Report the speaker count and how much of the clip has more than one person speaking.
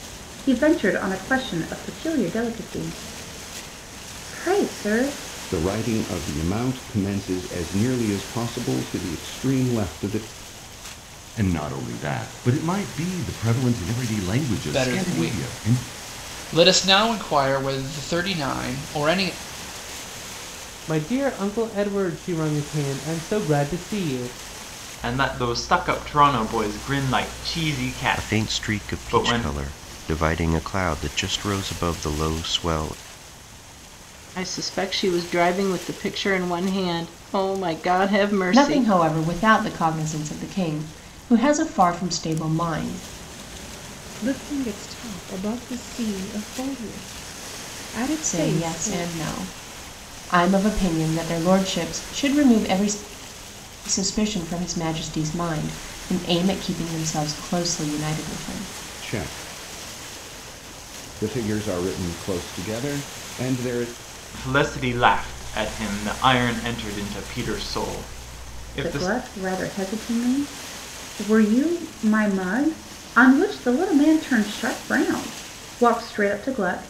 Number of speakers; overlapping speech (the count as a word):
ten, about 5%